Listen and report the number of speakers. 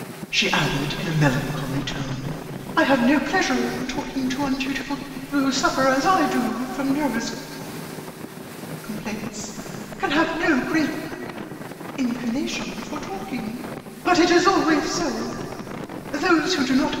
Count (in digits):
1